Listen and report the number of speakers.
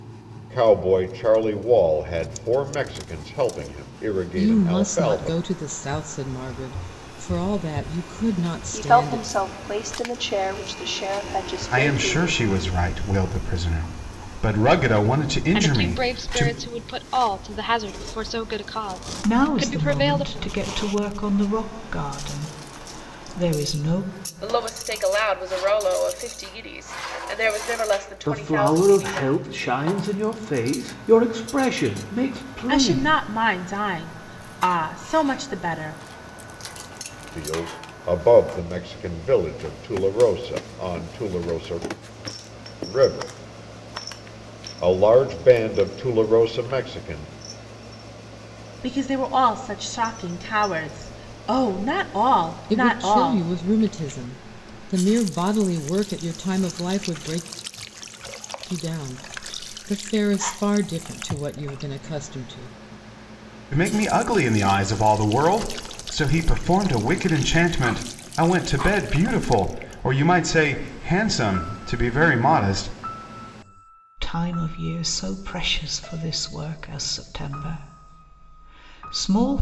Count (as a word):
nine